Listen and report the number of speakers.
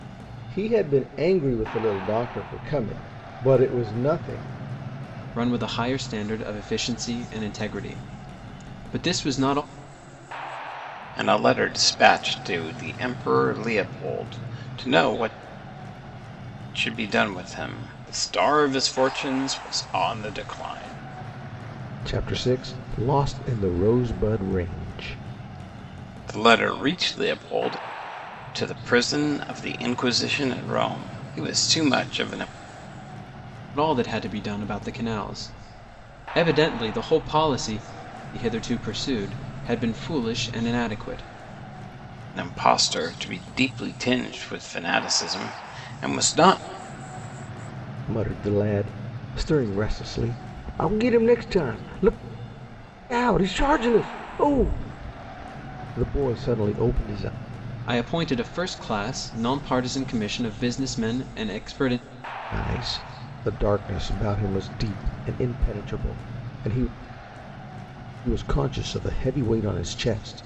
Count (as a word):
three